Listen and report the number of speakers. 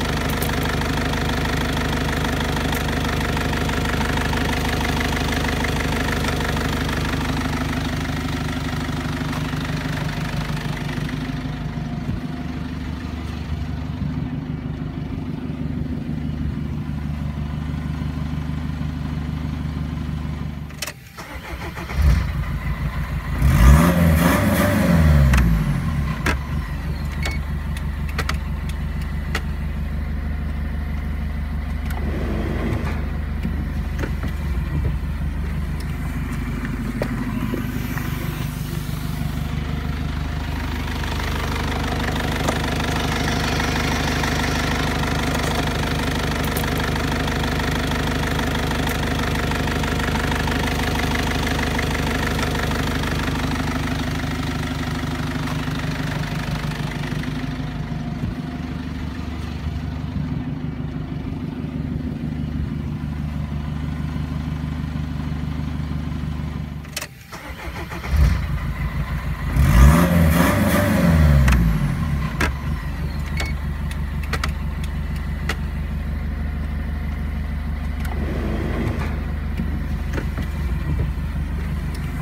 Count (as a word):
zero